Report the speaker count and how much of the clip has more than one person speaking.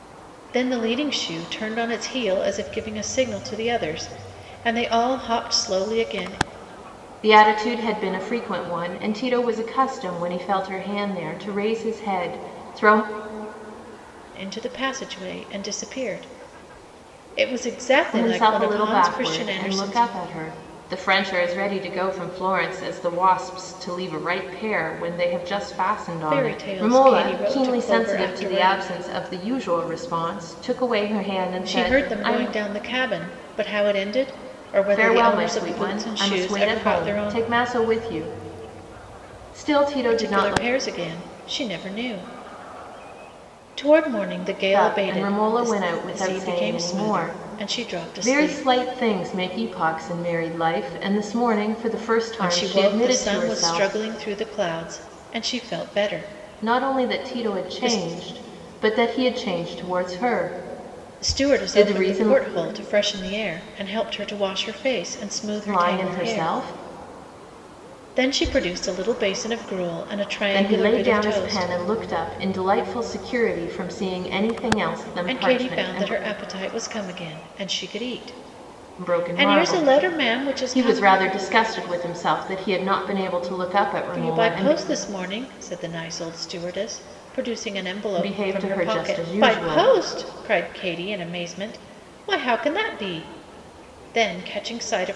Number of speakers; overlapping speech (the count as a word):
two, about 25%